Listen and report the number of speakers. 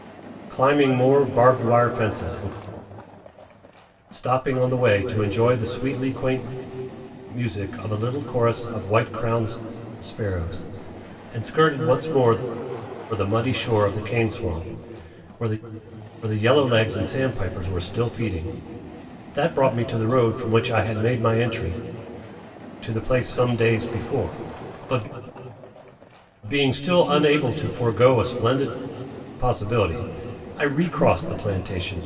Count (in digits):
1